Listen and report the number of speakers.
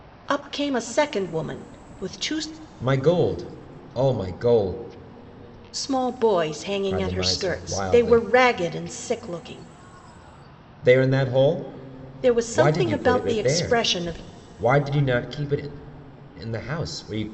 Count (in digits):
2